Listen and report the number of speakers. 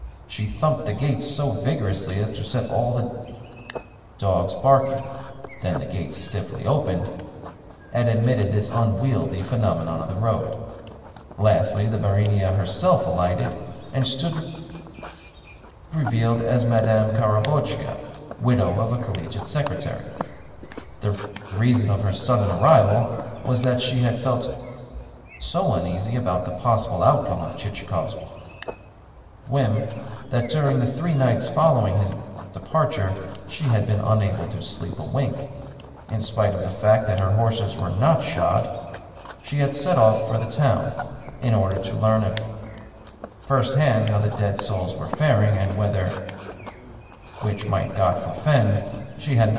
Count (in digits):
1